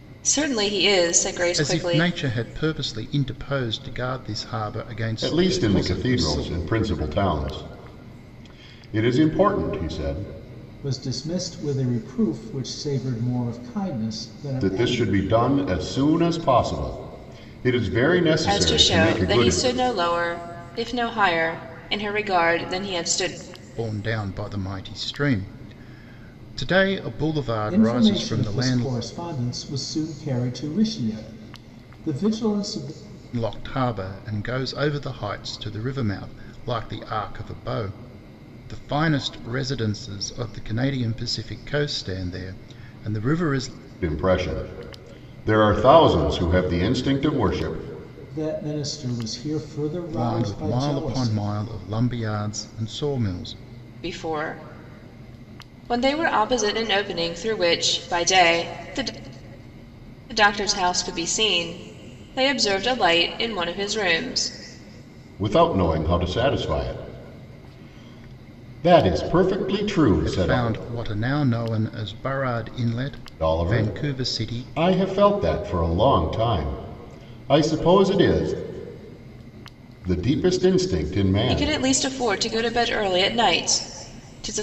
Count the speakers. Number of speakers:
four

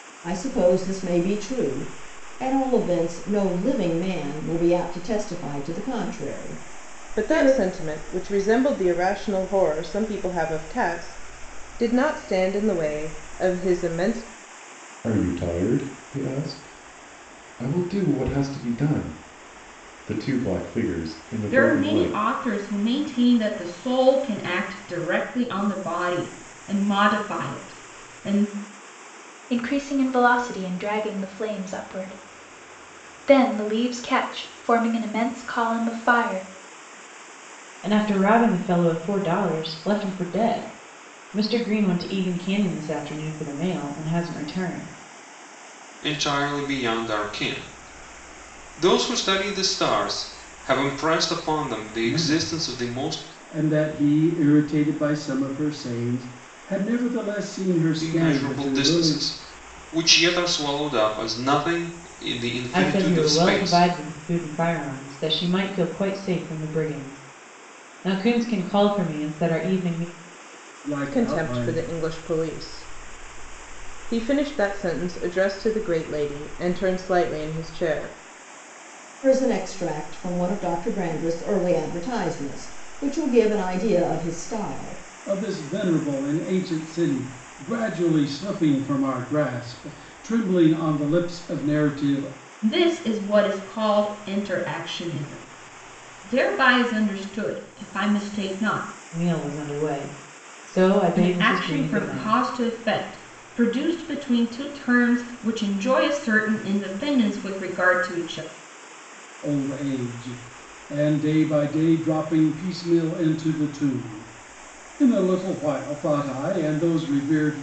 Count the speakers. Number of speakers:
eight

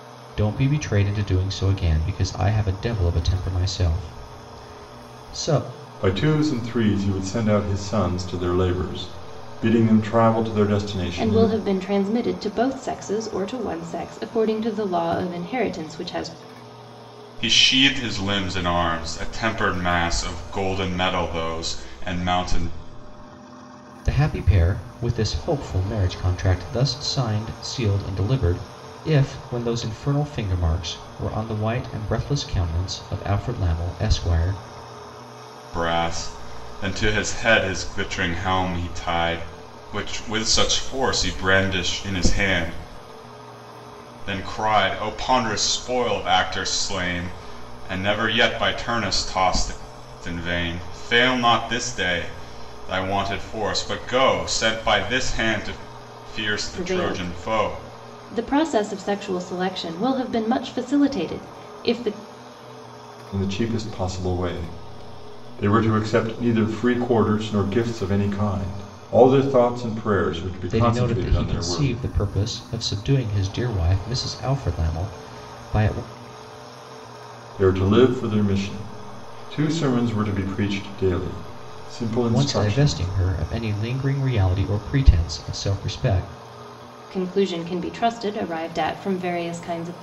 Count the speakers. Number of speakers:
four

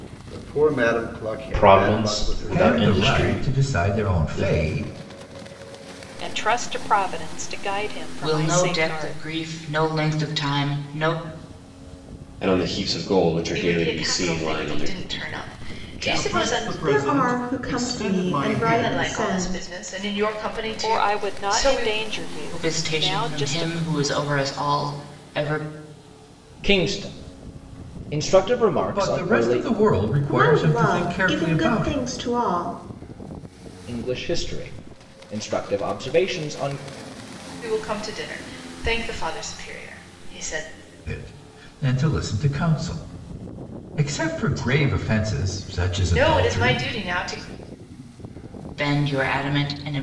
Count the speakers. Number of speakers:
ten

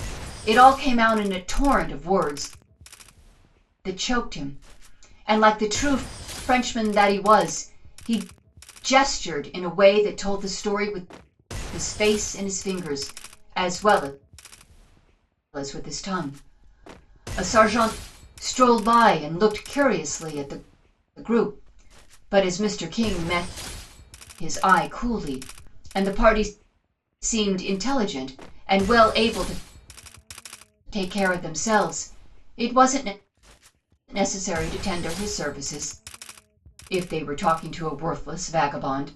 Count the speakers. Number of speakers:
one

